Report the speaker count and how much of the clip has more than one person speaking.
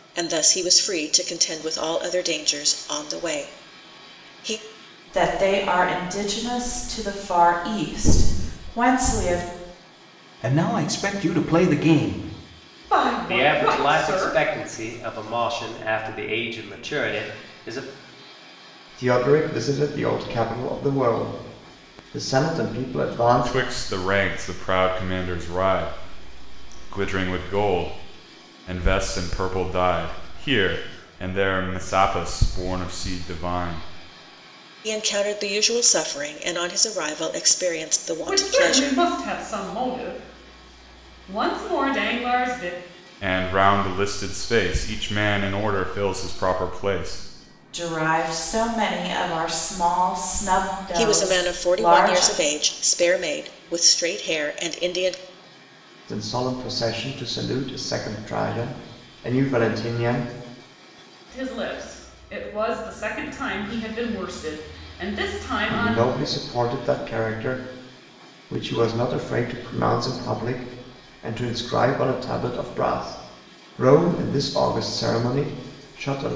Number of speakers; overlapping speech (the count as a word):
seven, about 5%